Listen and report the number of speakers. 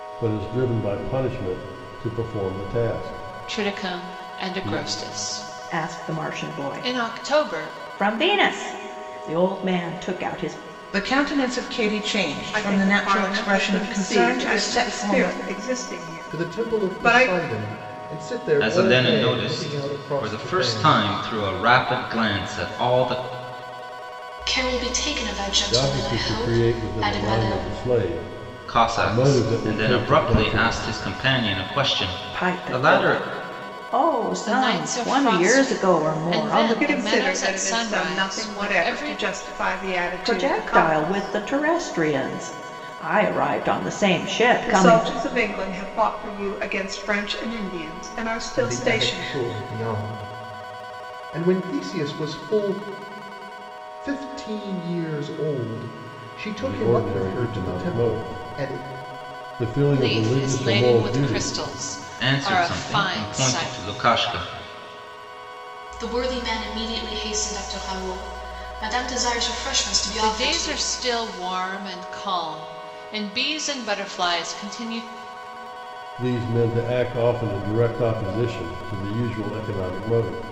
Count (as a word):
eight